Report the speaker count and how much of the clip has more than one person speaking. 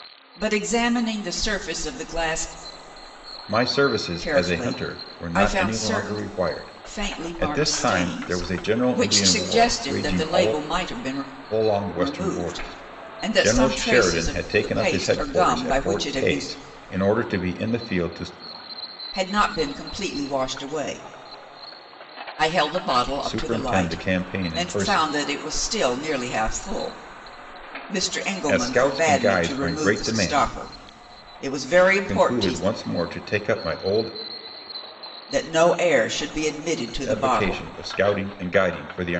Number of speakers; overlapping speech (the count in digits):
2, about 40%